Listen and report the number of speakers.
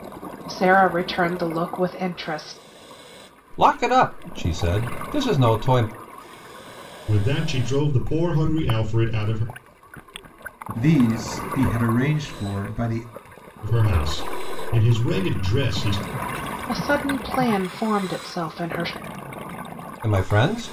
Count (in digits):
4